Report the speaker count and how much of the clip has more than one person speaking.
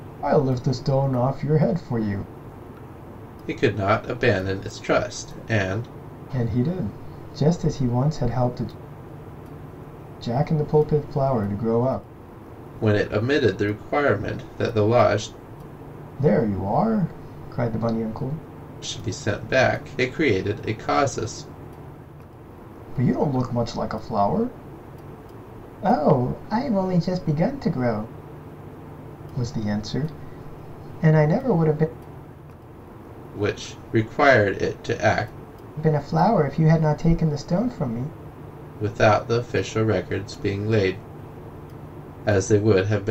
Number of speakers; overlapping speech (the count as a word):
two, no overlap